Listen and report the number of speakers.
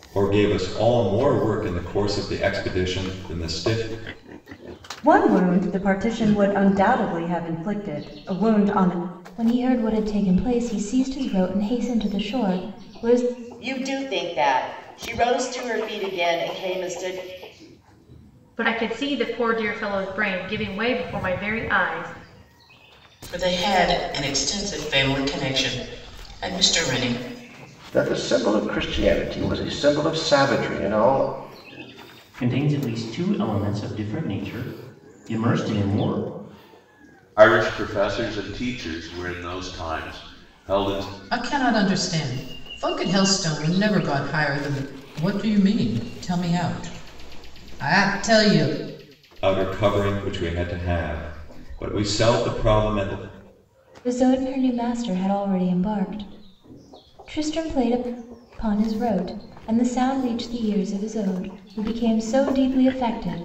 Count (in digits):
10